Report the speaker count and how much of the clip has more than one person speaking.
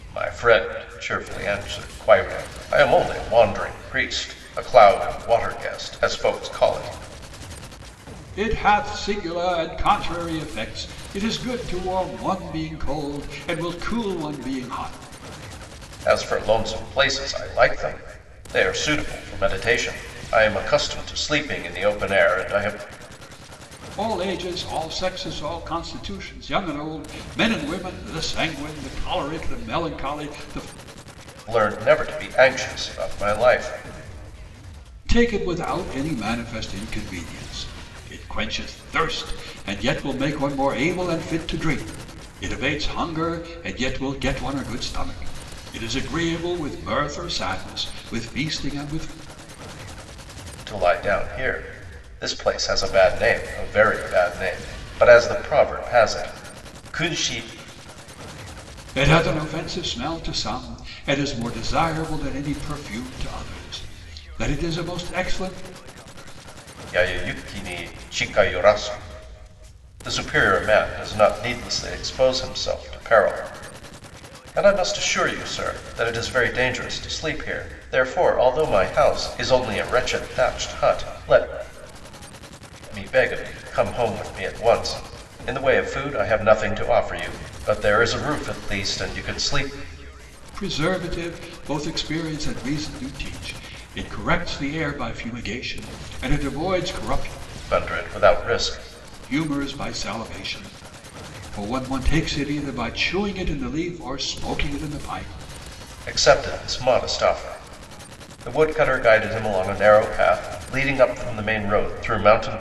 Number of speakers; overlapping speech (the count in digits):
2, no overlap